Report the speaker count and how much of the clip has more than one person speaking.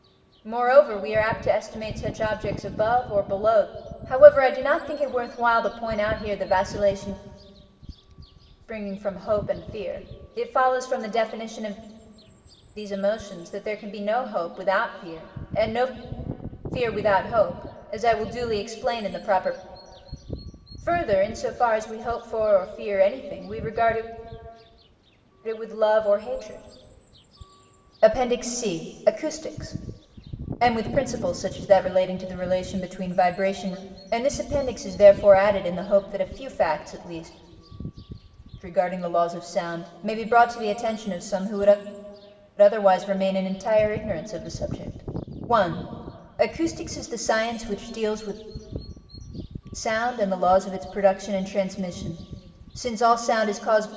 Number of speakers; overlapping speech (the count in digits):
1, no overlap